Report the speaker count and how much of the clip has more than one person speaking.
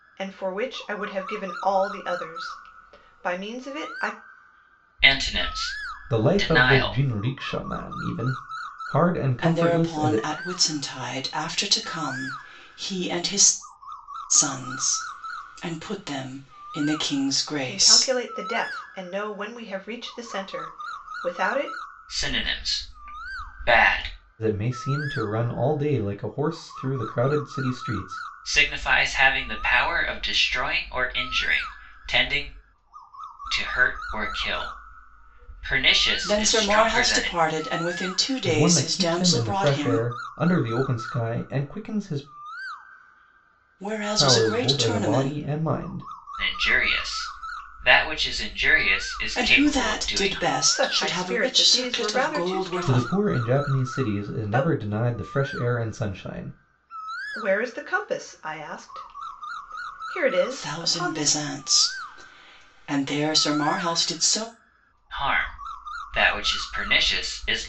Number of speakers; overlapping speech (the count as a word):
four, about 18%